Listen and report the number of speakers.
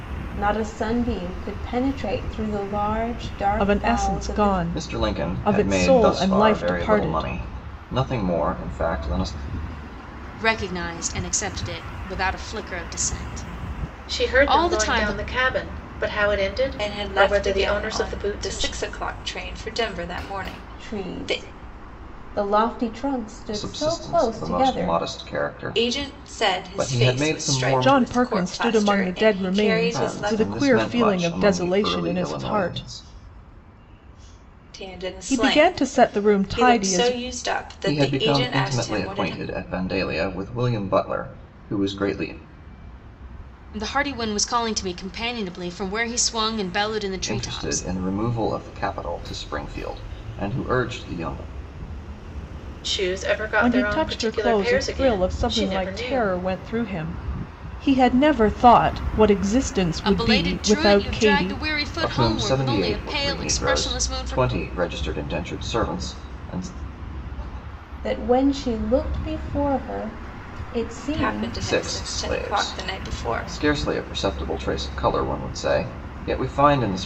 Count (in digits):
6